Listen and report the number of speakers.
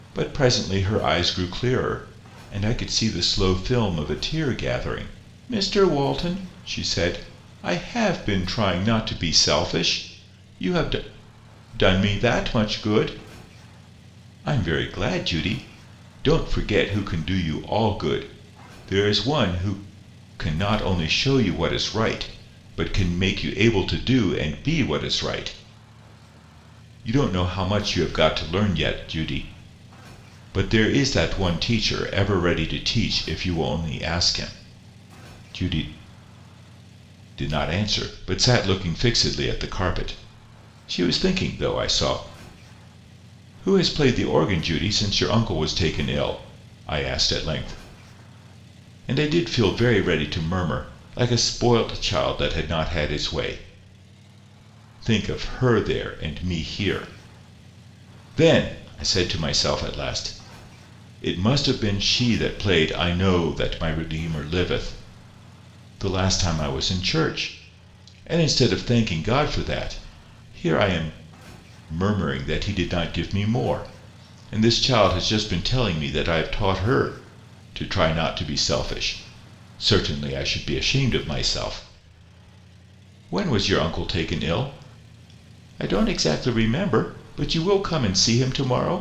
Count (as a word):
one